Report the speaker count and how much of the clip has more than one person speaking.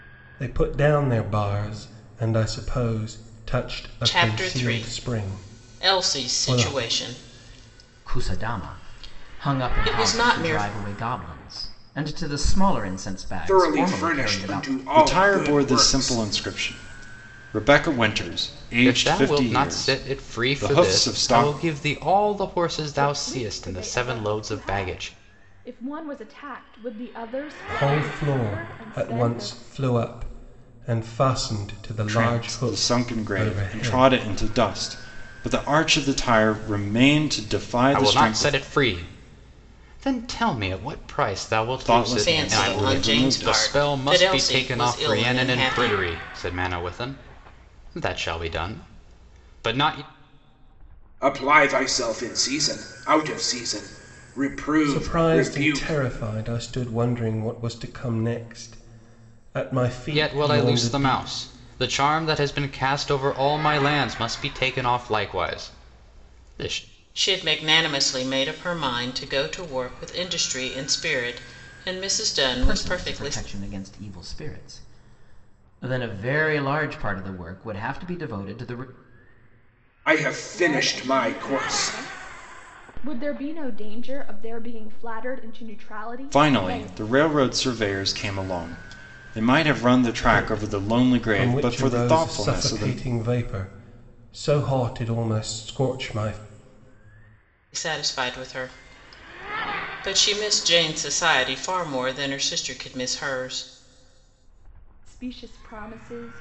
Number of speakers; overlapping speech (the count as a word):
seven, about 29%